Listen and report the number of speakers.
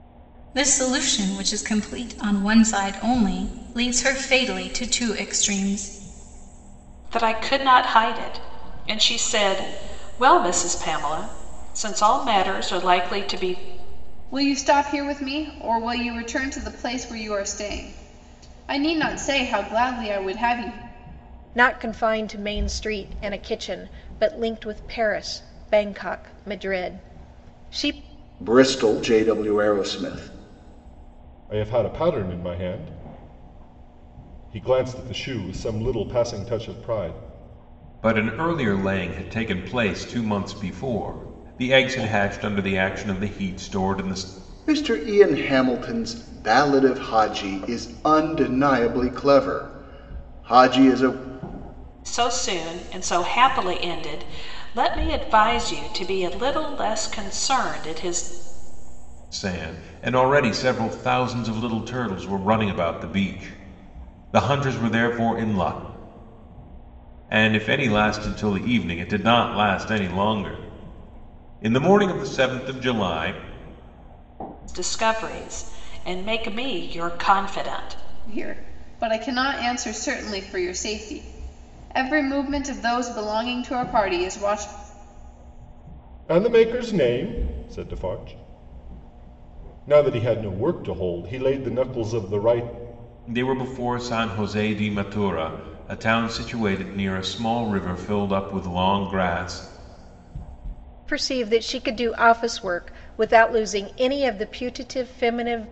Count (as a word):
seven